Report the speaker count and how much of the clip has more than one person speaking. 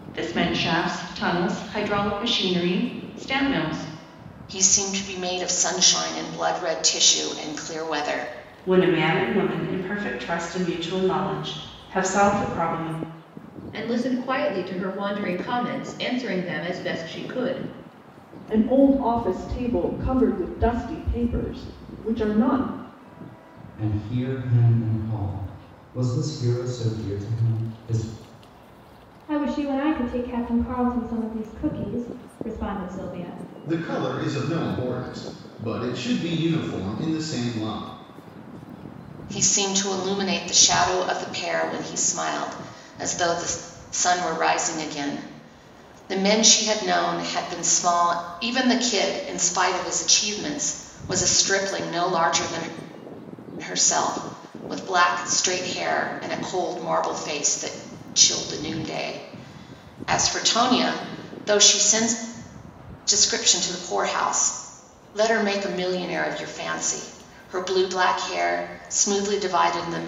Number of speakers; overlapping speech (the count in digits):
8, no overlap